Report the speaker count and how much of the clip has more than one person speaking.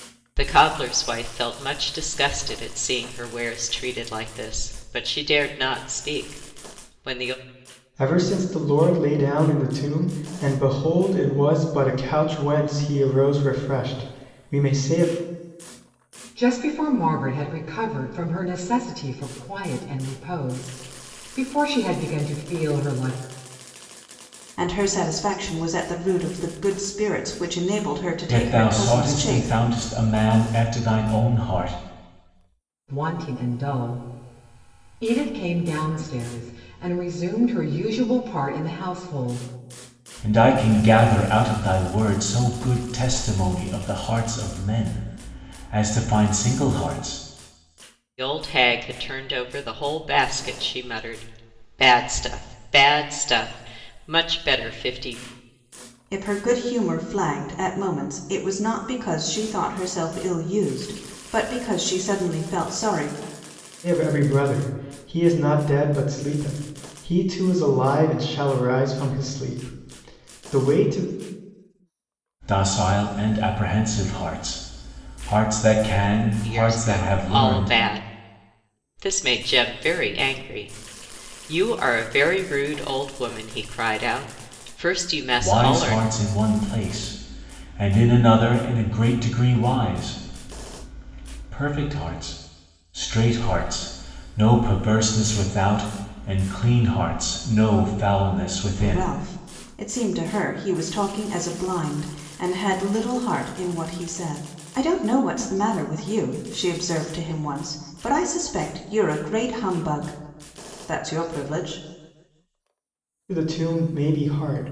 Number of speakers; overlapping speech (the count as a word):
five, about 3%